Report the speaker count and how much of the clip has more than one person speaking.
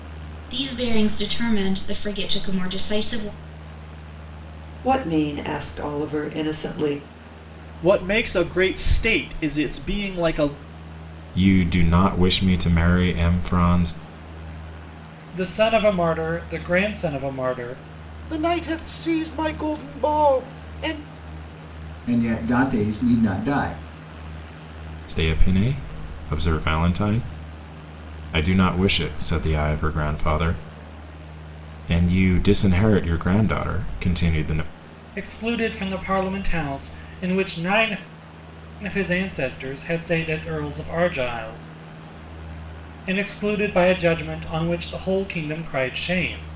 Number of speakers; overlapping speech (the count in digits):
7, no overlap